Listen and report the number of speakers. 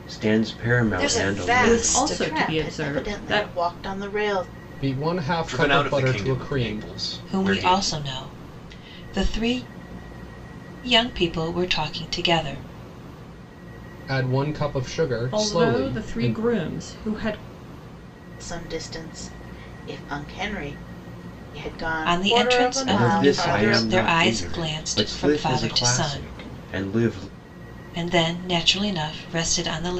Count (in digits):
7